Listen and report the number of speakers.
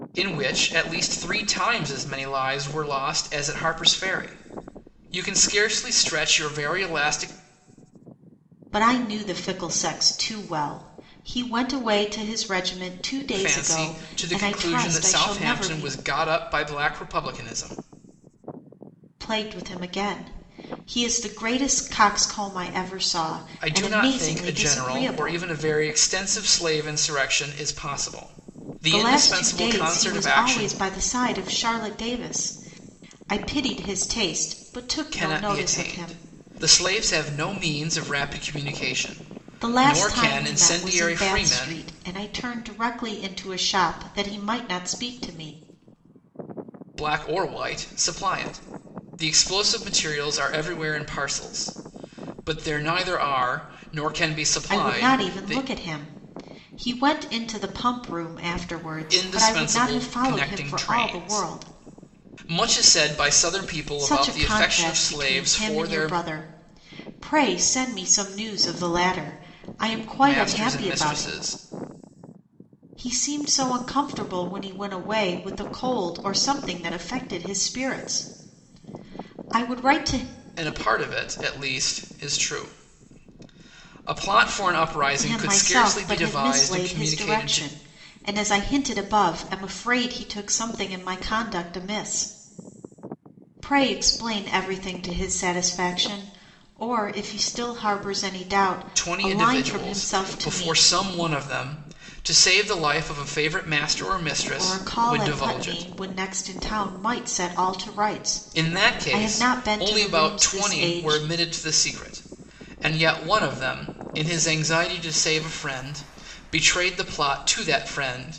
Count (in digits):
2